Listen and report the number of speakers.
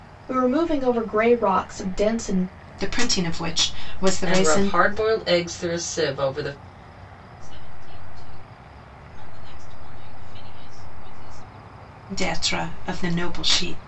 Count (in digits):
4